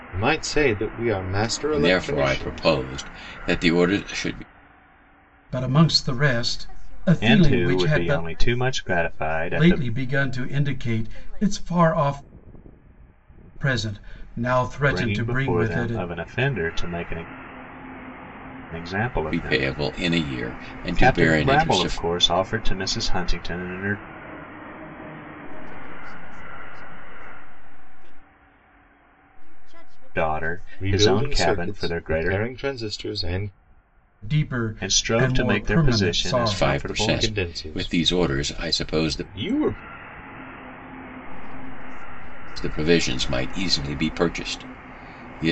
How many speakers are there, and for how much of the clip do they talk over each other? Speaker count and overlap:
5, about 42%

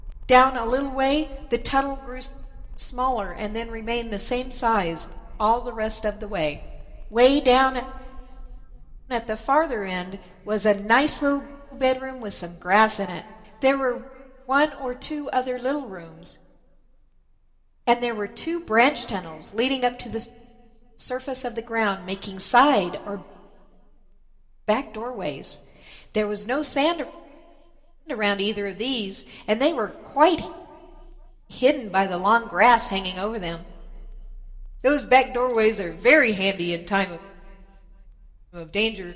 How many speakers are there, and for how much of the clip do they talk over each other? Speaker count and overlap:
1, no overlap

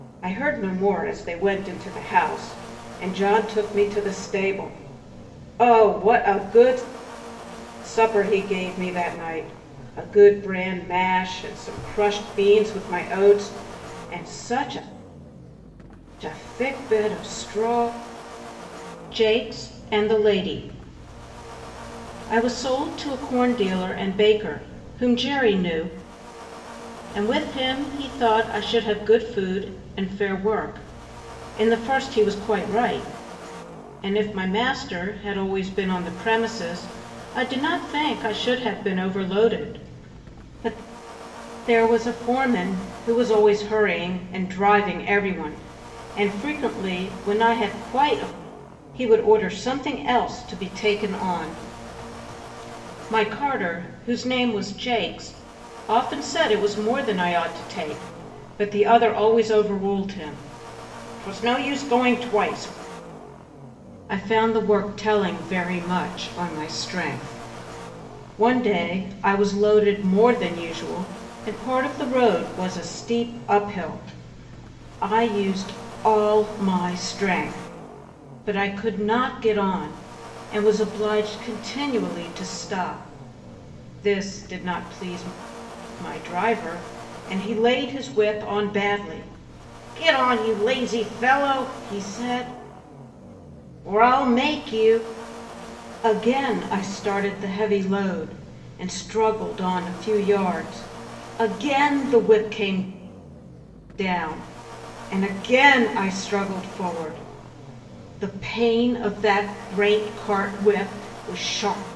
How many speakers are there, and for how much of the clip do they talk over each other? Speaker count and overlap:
1, no overlap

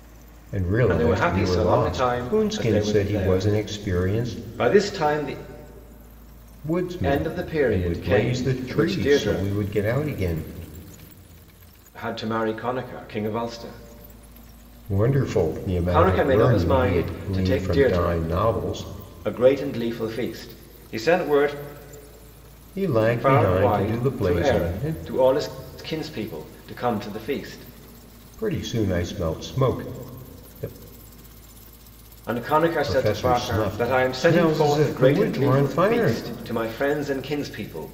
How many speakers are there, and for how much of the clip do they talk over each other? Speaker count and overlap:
2, about 36%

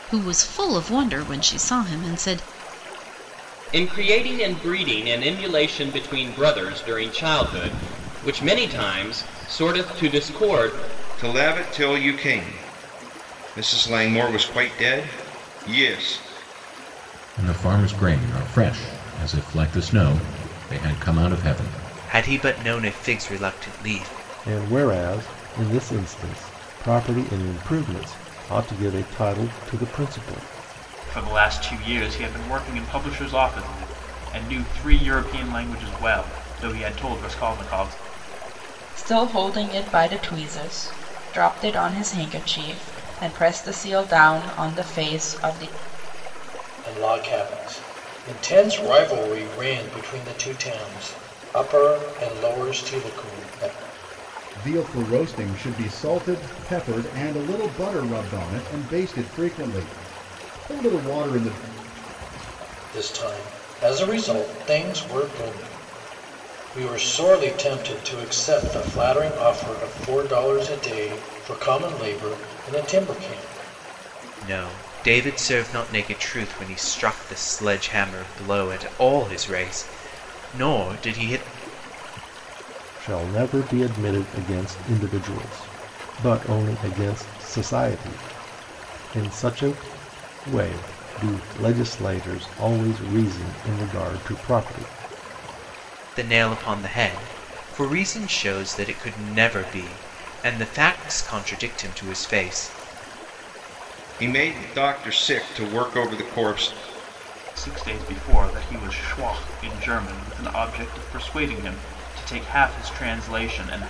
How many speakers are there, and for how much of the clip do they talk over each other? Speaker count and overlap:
10, no overlap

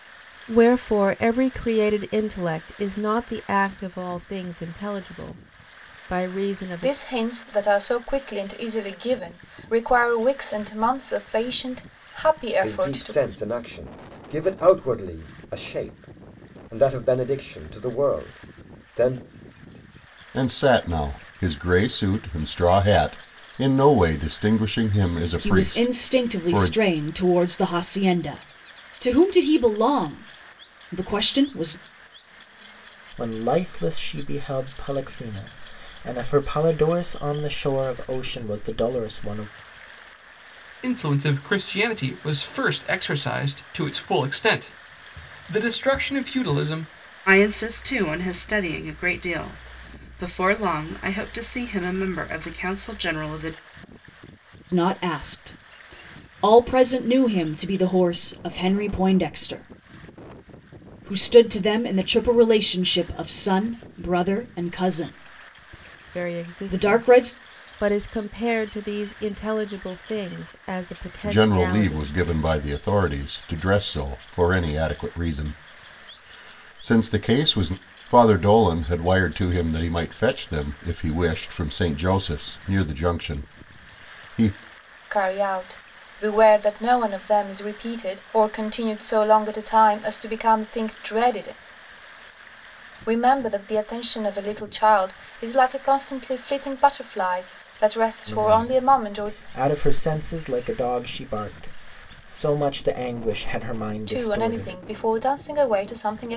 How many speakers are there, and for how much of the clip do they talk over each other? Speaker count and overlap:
8, about 6%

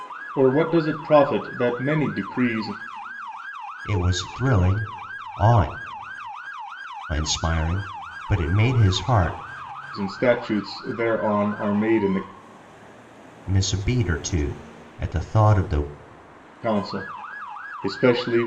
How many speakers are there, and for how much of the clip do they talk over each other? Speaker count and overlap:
2, no overlap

